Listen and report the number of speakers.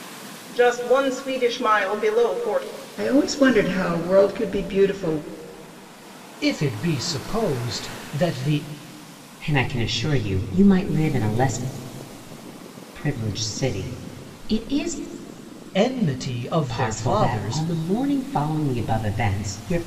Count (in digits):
4